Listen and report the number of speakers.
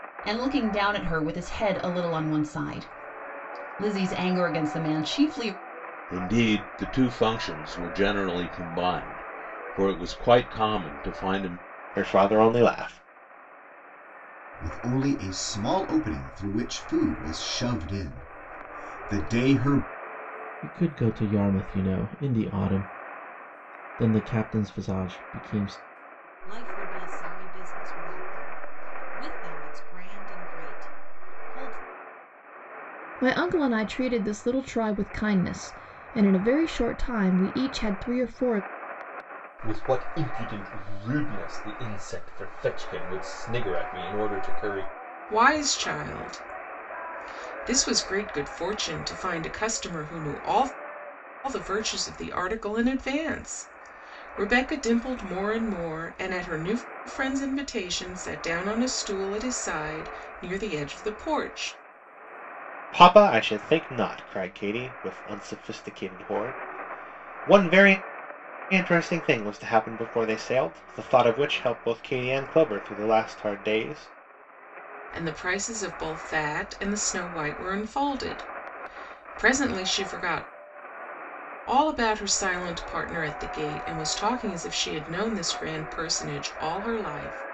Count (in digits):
9